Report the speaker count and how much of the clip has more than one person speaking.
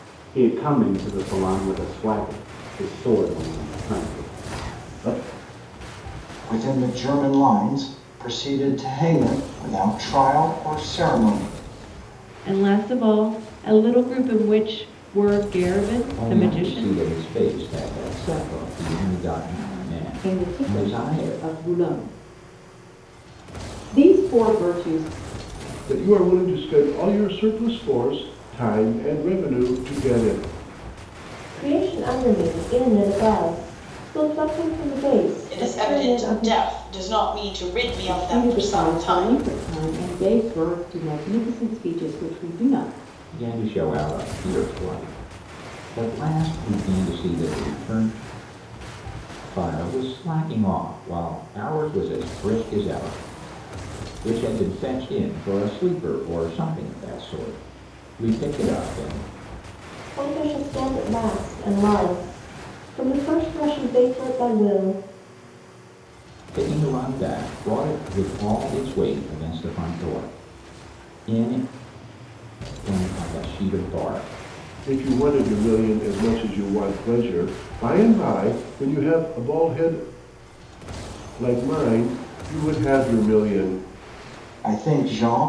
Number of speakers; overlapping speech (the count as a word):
eight, about 5%